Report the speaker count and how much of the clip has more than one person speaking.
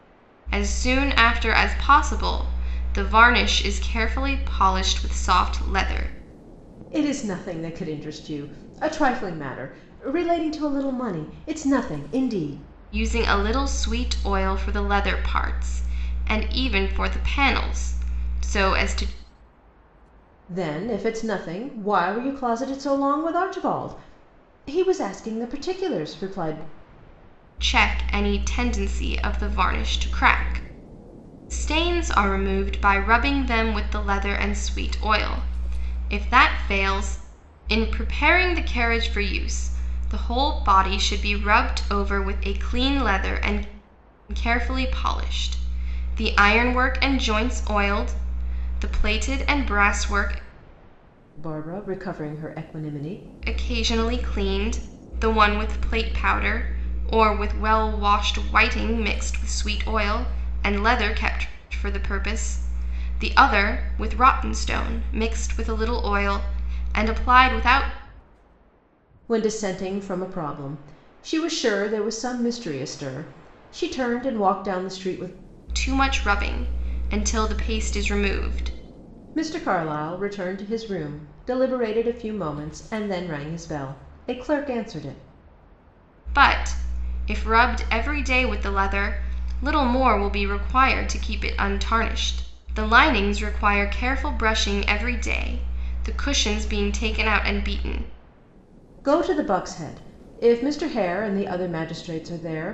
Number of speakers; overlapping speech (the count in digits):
2, no overlap